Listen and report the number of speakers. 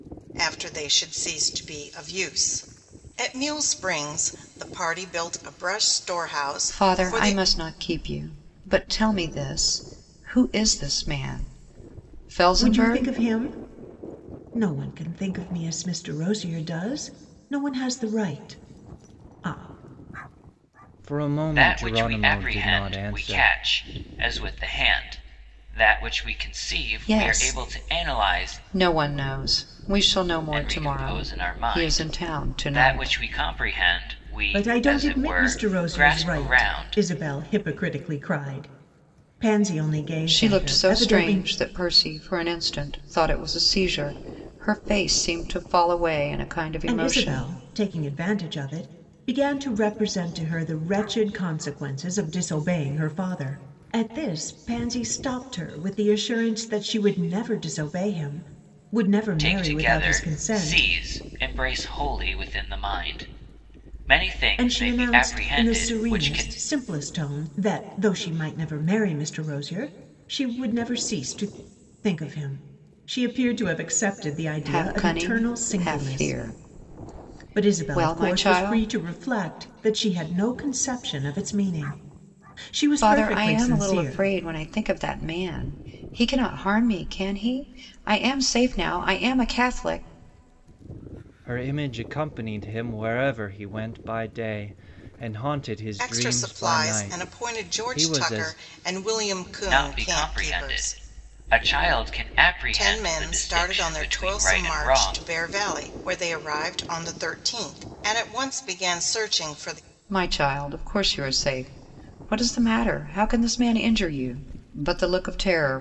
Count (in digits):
5